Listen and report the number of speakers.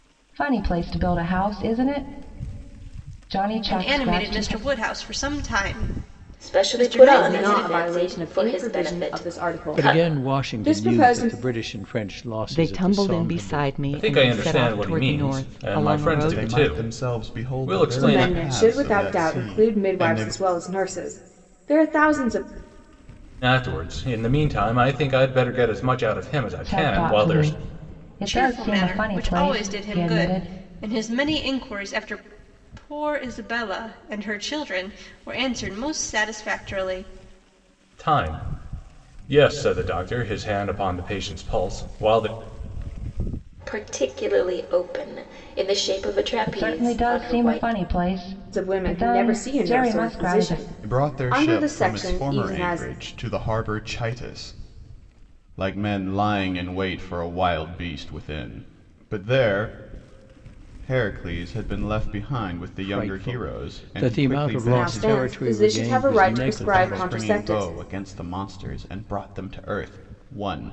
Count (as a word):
eight